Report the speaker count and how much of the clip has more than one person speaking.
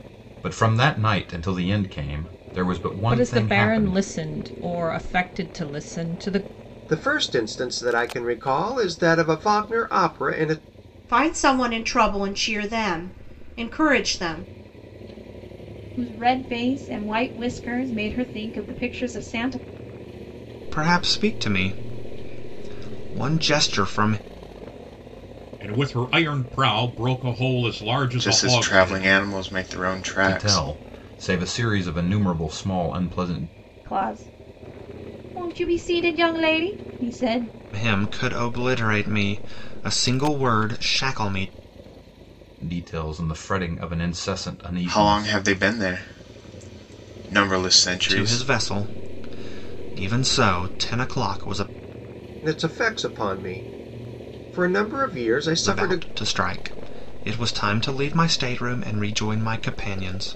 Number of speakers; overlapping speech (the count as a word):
eight, about 7%